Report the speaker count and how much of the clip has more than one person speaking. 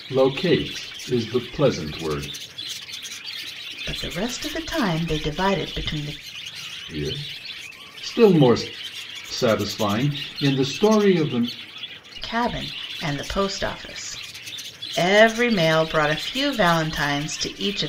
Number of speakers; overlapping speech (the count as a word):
two, no overlap